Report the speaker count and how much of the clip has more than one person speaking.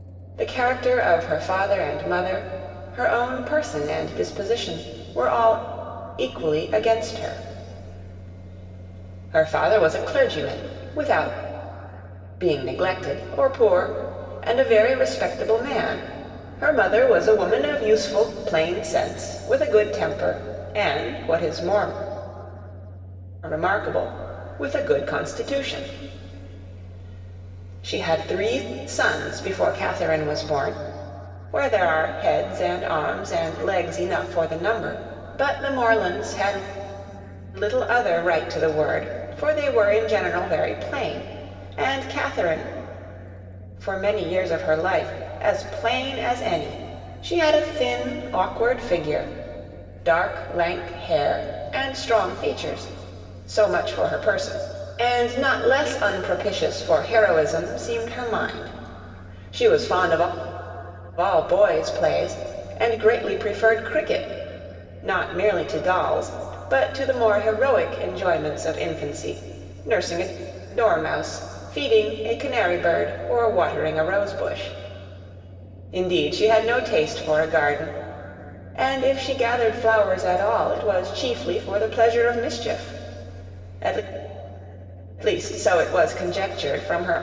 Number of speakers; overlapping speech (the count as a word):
one, no overlap